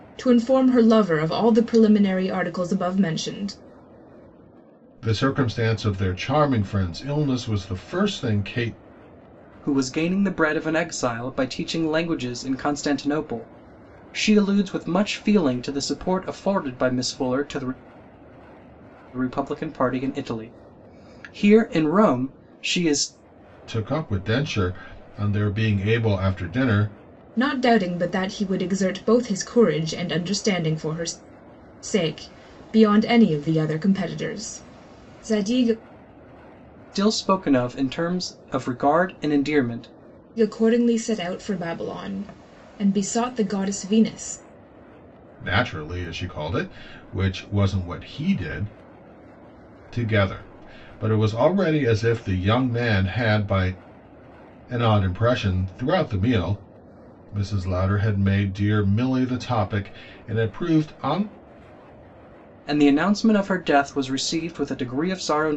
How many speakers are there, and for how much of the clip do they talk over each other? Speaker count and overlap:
3, no overlap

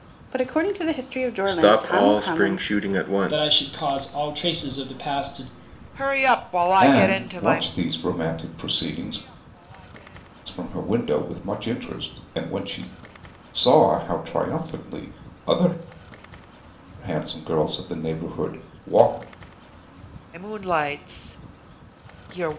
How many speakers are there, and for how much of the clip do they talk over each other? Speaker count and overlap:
5, about 11%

